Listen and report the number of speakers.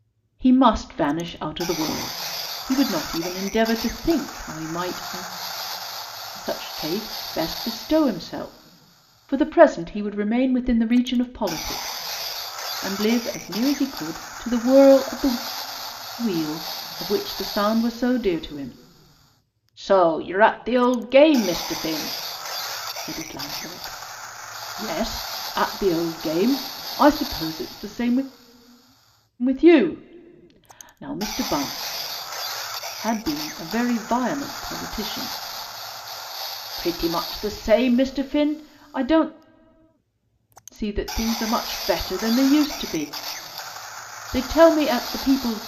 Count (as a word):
one